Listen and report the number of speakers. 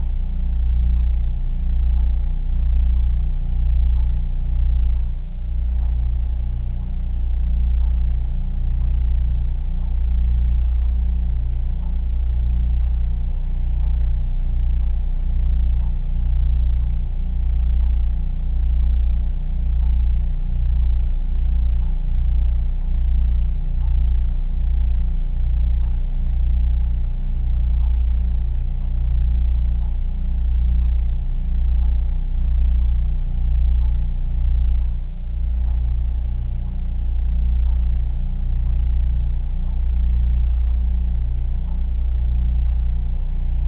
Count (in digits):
0